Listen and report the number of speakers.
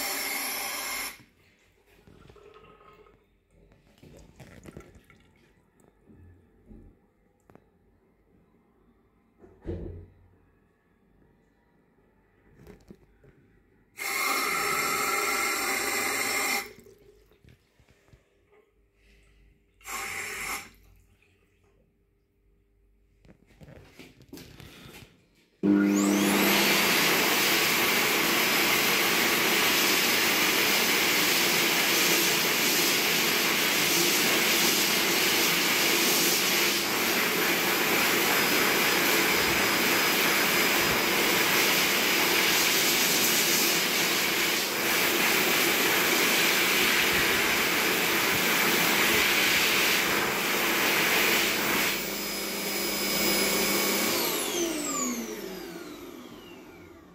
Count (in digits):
0